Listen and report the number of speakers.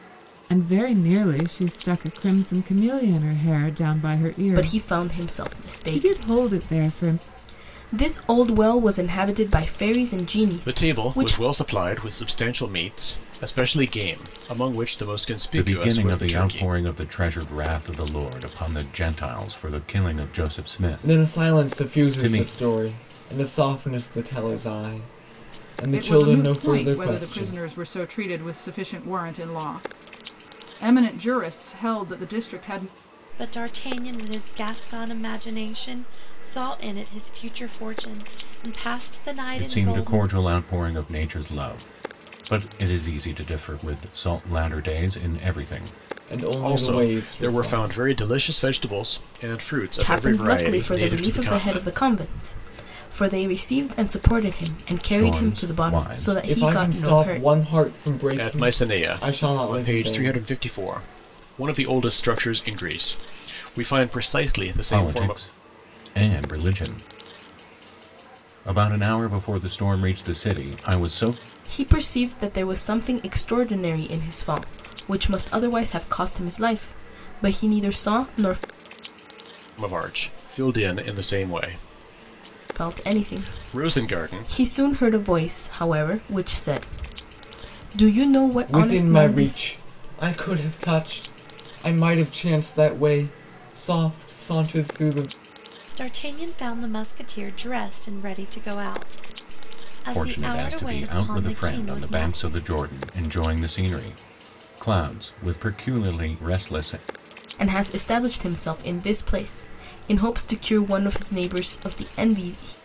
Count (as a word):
seven